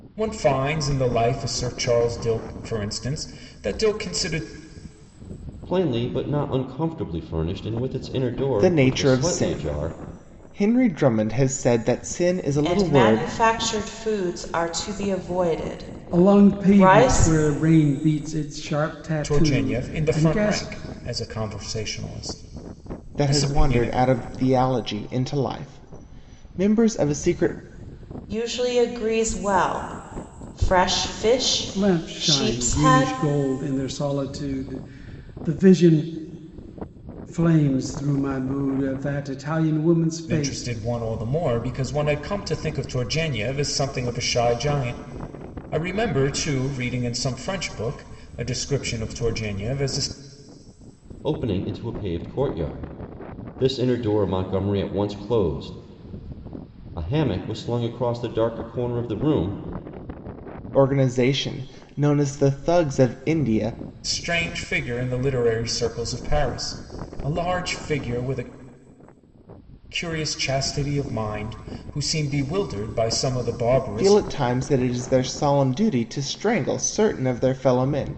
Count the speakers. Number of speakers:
5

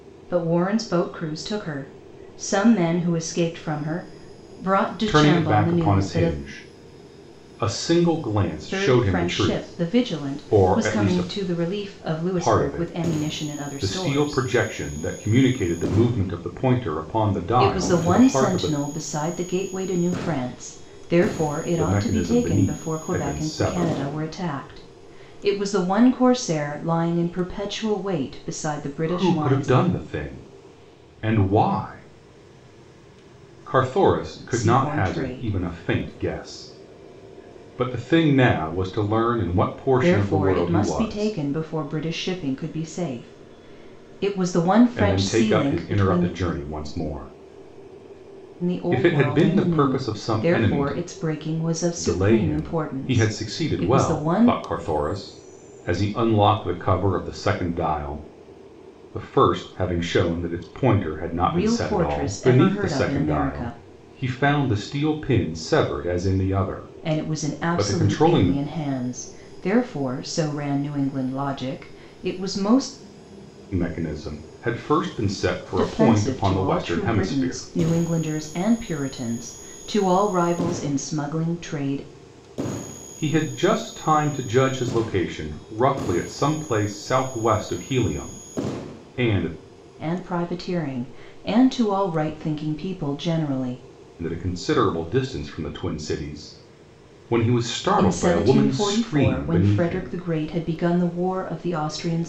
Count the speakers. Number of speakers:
2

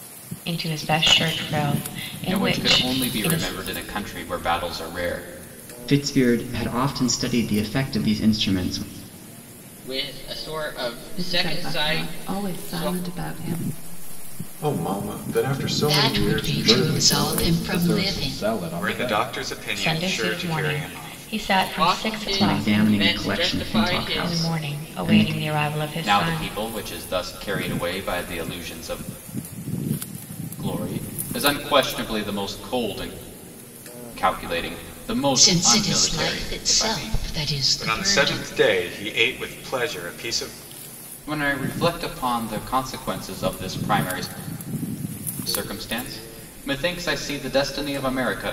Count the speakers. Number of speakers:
9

